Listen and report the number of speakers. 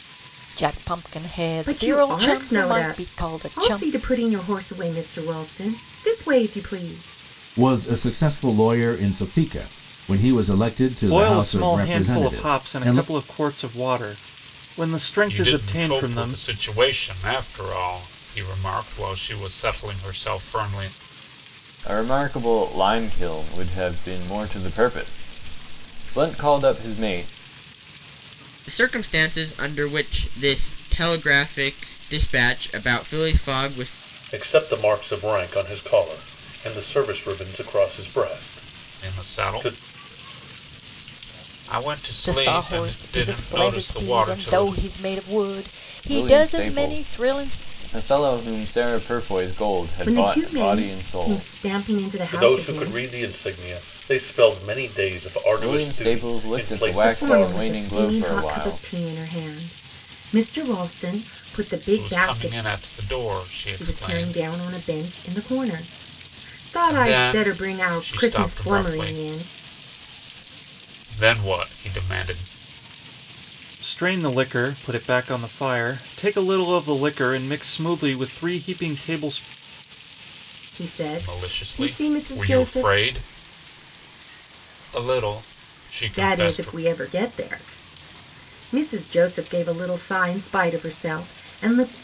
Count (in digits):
8